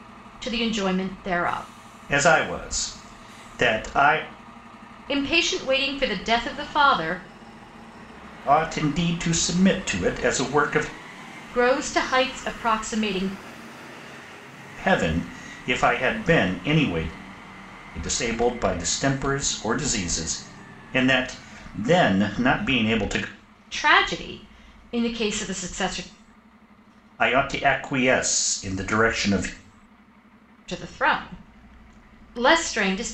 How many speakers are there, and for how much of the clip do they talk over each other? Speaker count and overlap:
2, no overlap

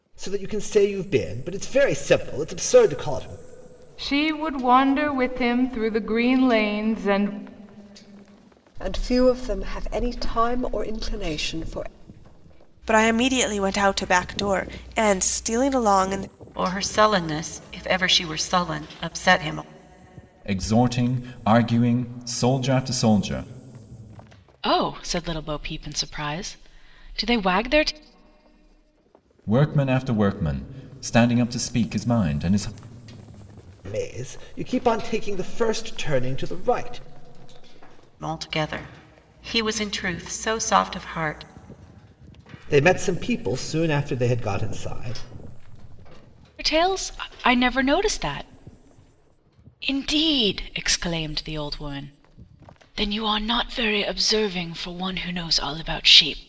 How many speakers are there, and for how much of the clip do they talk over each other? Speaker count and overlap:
7, no overlap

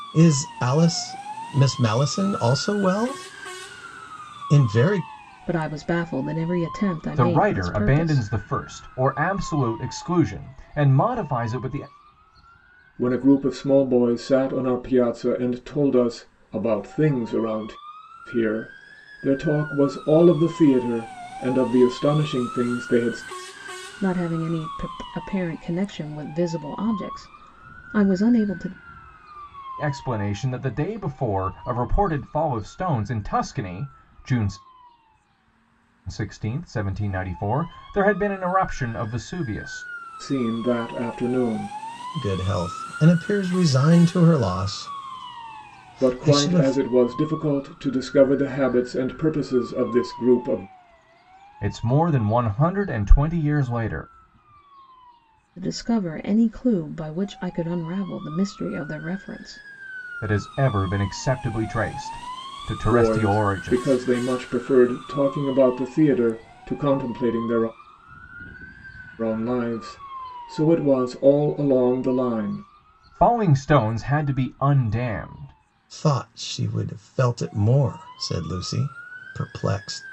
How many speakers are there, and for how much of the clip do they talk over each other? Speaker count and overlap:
4, about 4%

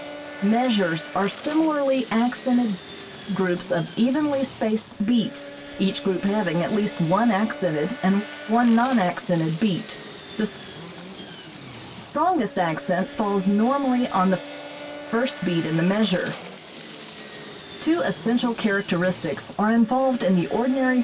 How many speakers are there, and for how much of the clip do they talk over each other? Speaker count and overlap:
1, no overlap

